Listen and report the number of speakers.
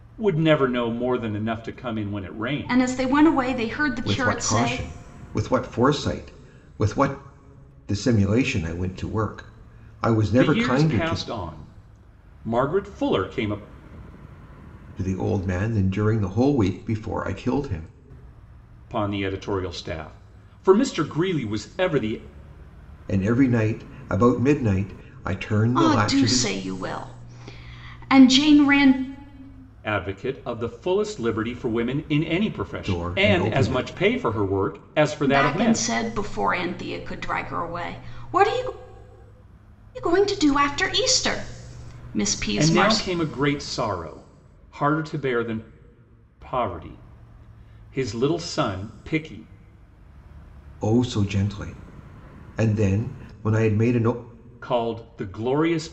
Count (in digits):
3